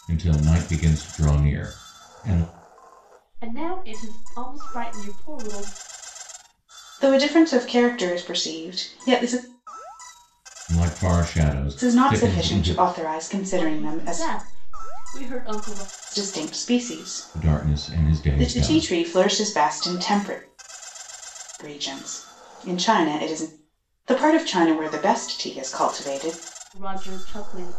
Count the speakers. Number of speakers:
three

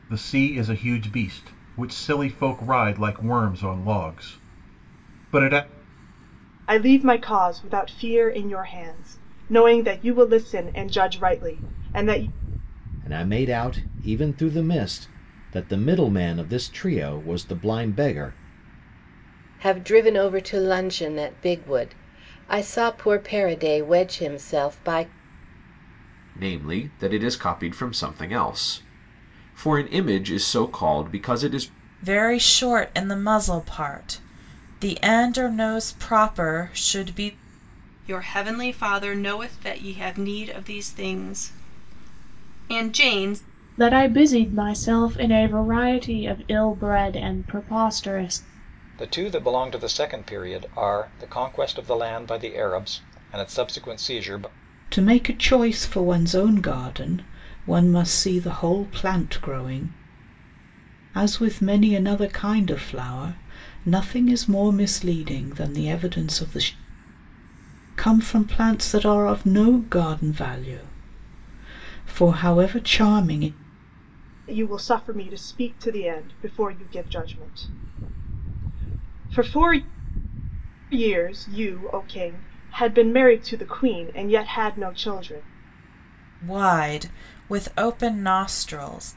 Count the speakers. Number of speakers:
ten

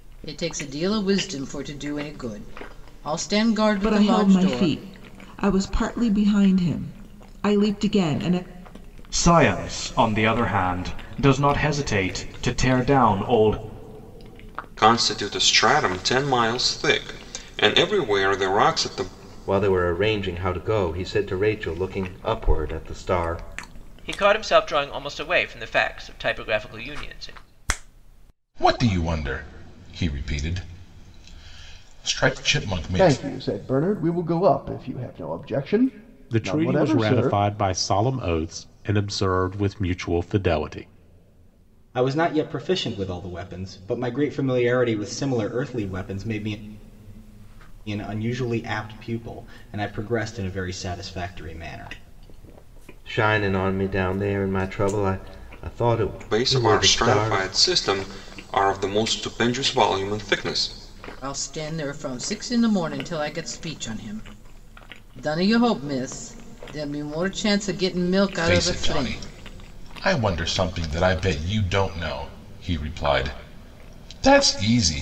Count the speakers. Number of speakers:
ten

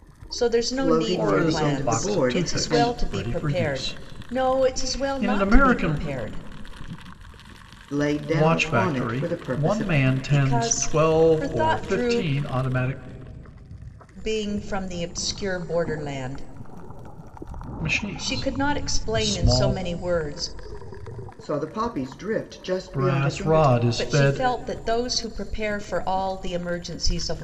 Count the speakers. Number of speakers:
three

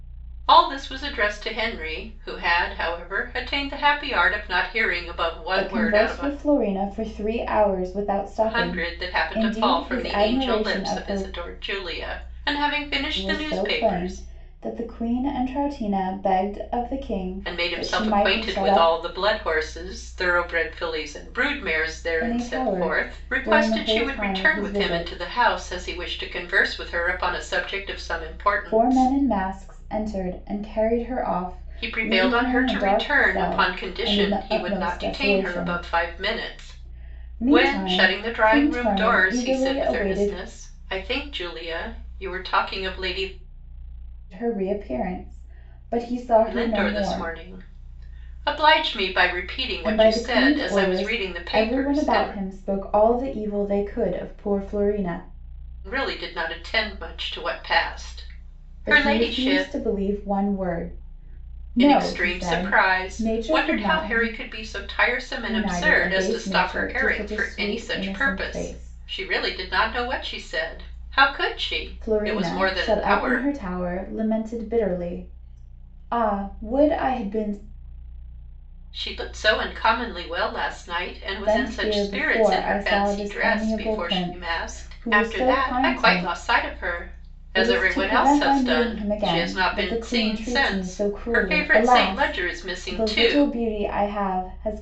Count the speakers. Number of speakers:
two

